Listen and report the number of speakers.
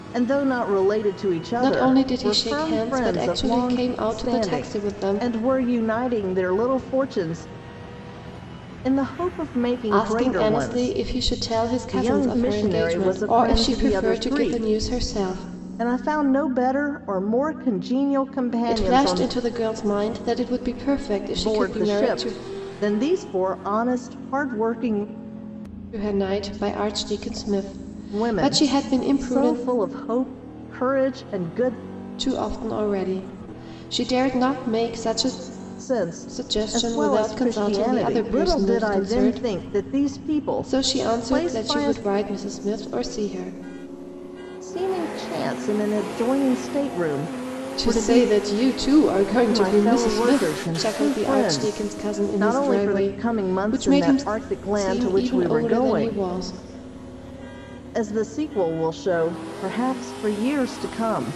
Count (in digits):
2